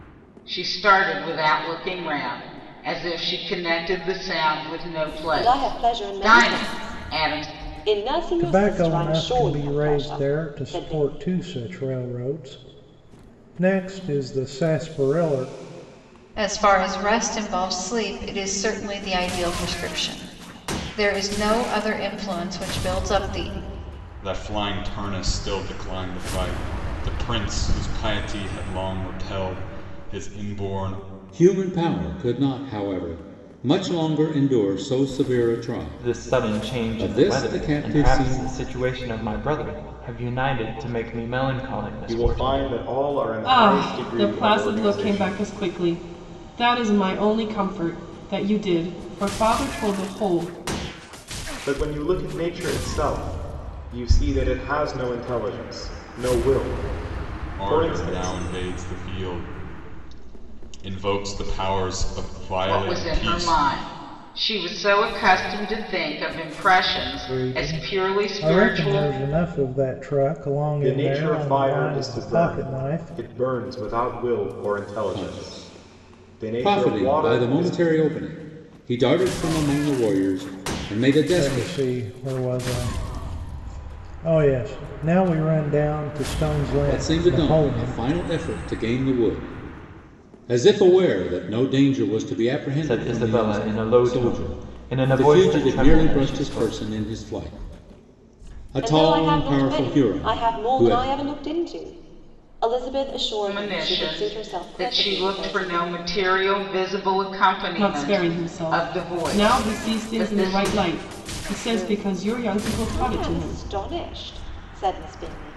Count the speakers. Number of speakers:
nine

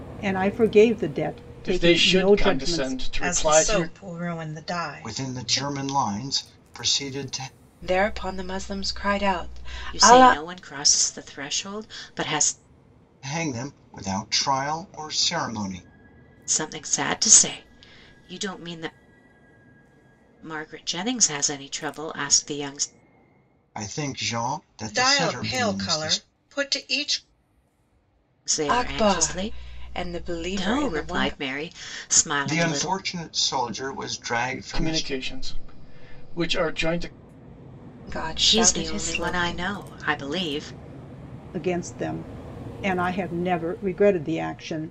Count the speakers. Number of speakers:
six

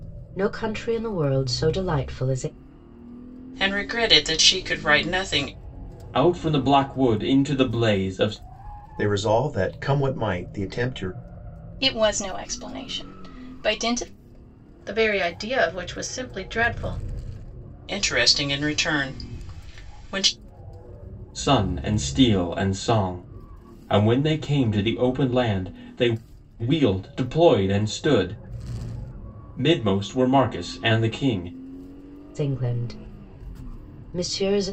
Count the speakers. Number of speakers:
six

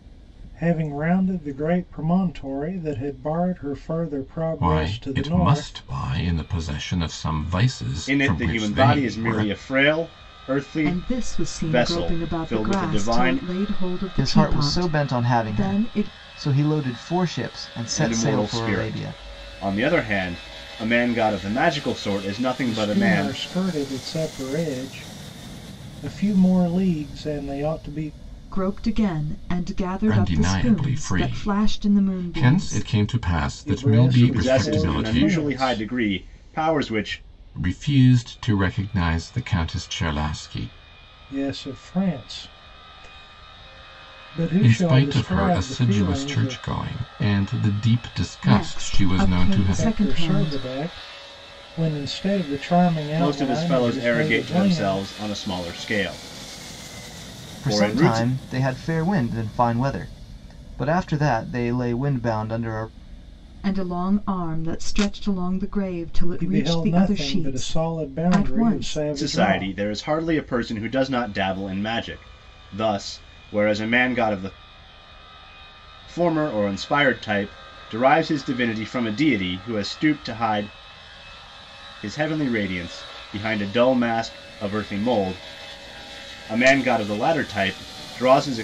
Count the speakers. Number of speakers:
five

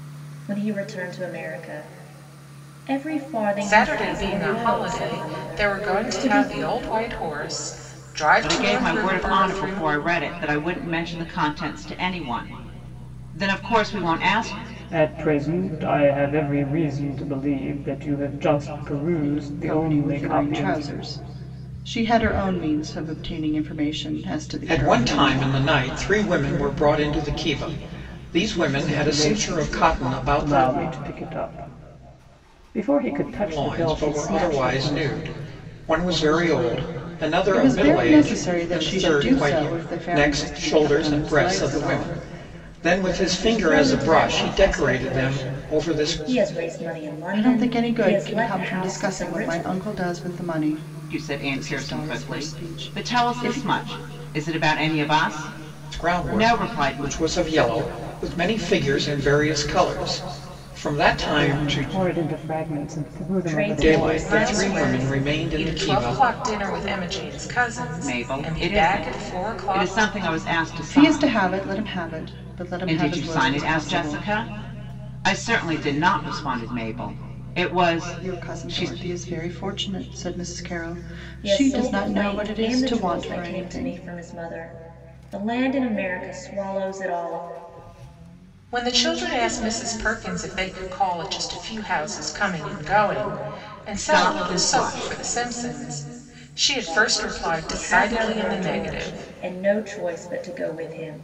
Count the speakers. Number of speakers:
six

